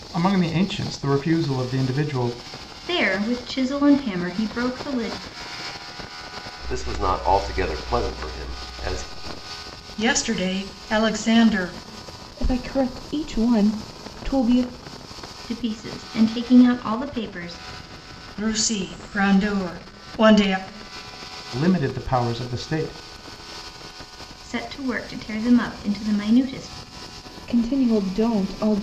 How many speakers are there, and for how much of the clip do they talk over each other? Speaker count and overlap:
five, no overlap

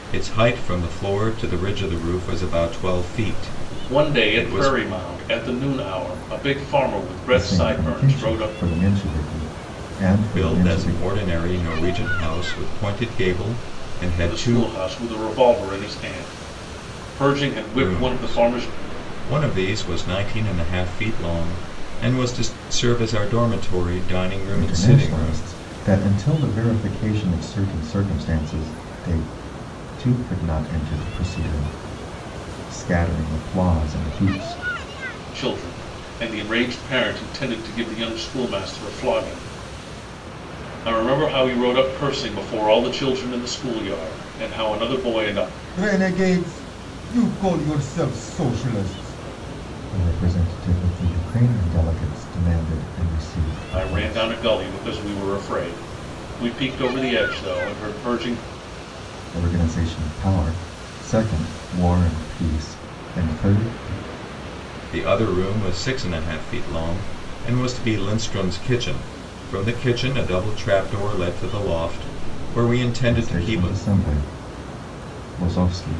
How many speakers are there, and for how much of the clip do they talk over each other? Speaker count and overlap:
three, about 9%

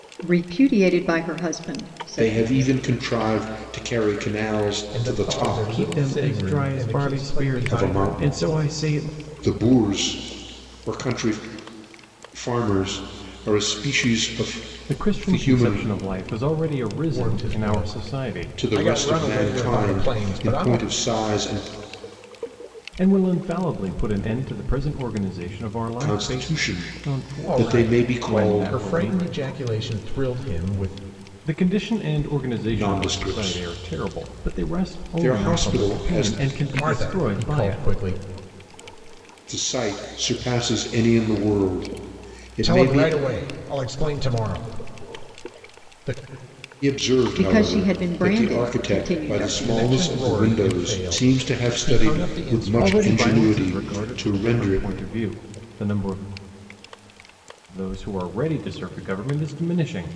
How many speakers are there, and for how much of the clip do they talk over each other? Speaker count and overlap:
four, about 42%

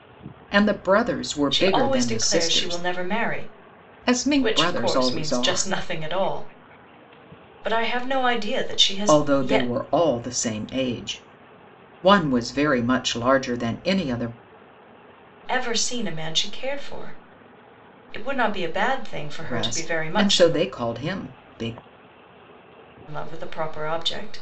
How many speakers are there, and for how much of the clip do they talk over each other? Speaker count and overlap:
two, about 19%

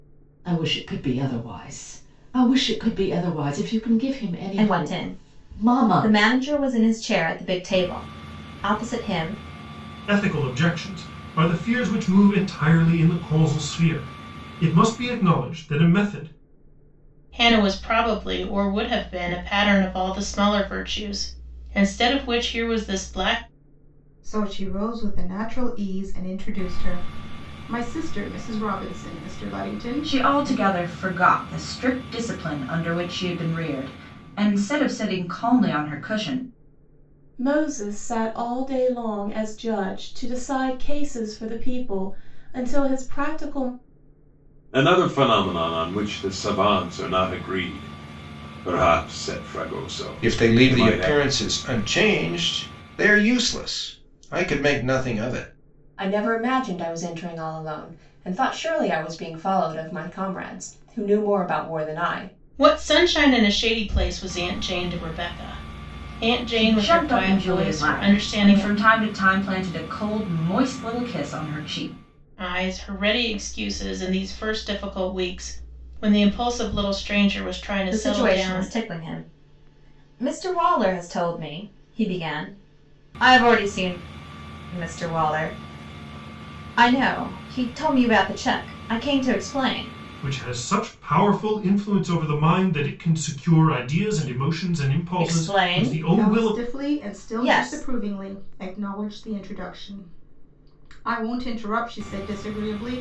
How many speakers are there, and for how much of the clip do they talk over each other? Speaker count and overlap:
ten, about 10%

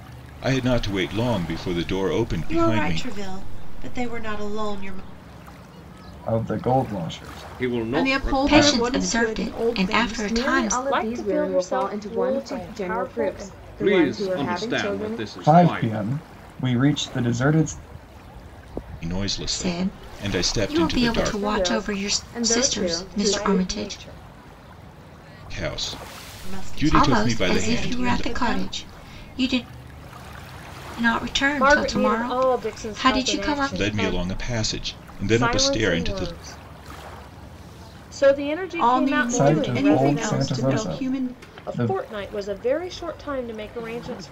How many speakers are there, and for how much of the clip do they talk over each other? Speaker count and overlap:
eight, about 50%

